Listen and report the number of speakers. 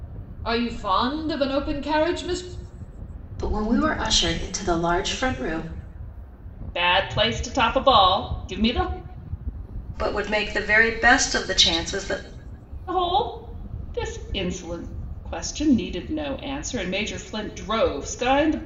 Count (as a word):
four